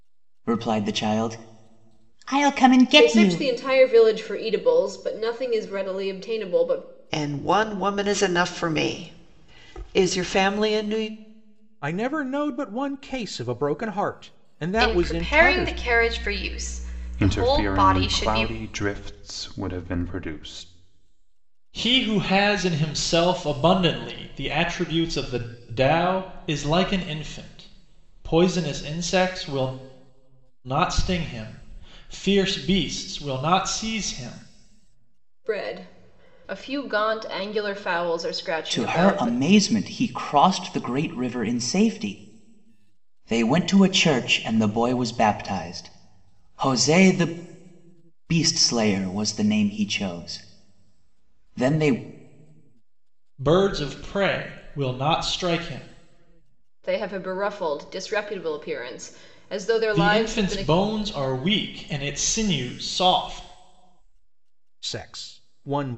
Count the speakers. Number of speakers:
seven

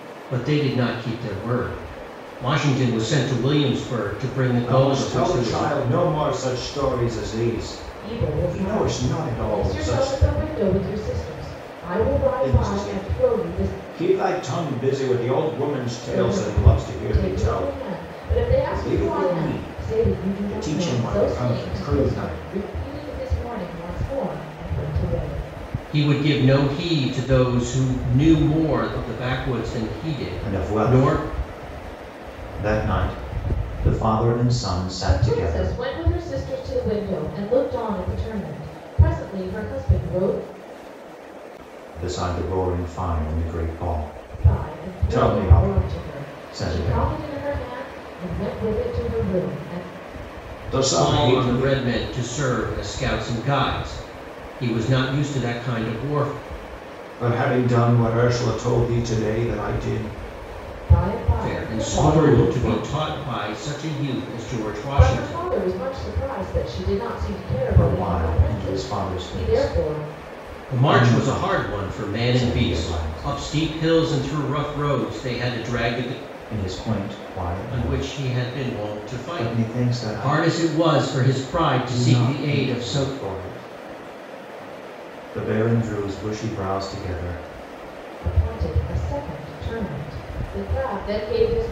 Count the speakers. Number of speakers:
three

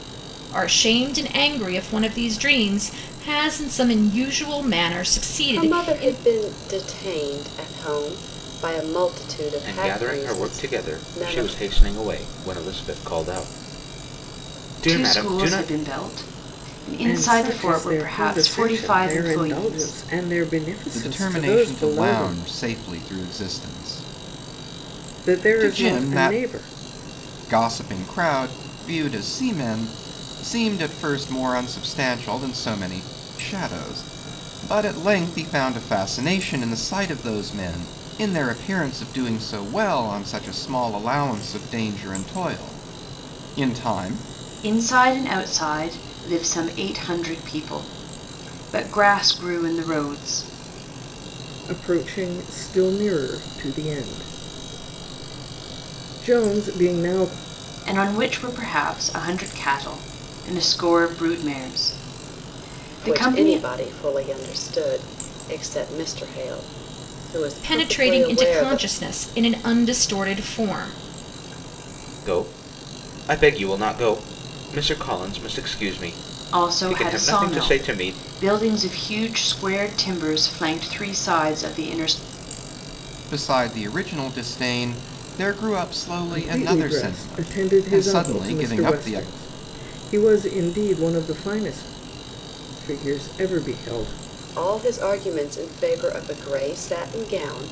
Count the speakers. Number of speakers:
six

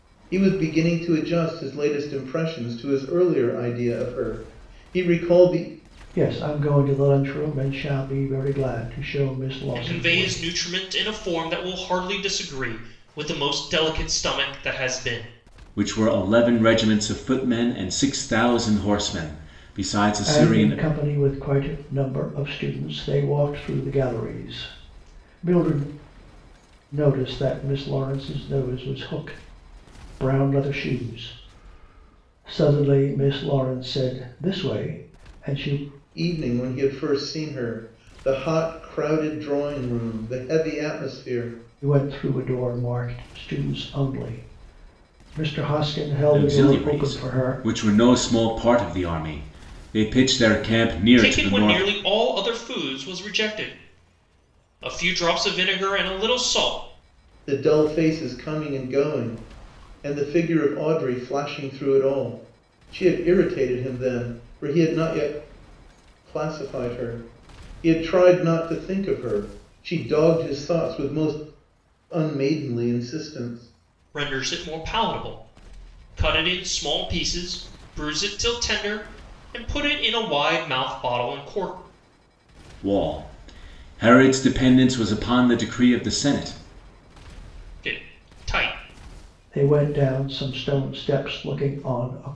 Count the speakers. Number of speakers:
four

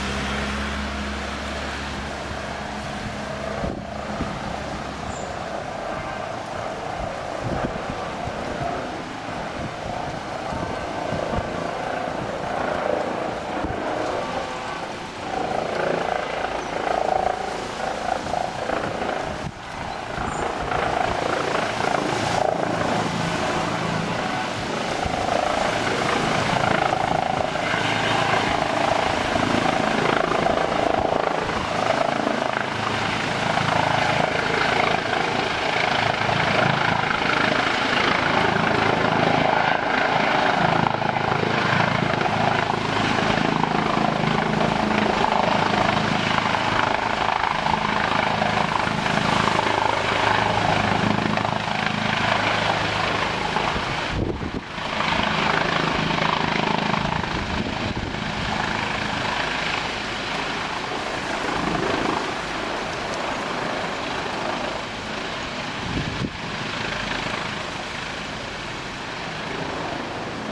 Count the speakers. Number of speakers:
zero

